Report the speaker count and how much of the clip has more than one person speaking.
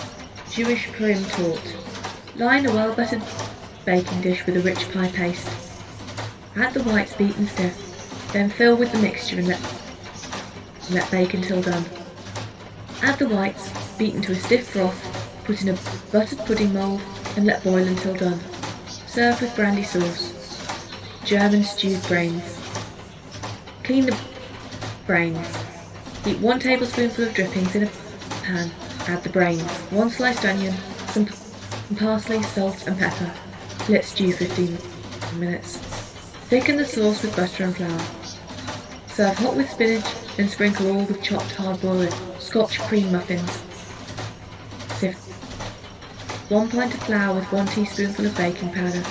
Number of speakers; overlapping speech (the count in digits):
1, no overlap